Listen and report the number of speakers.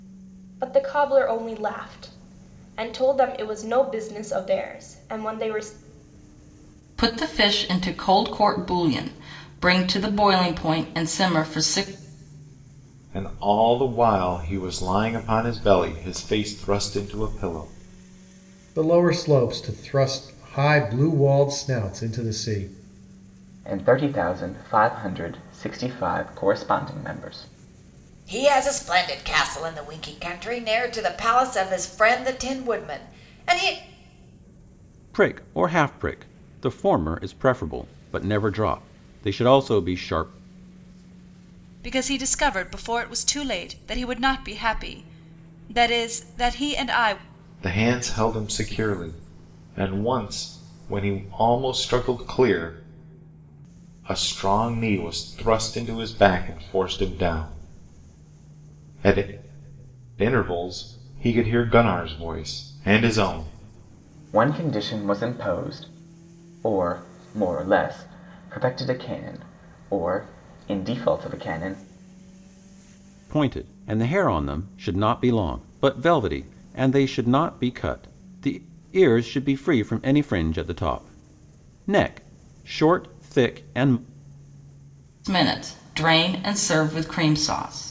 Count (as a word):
eight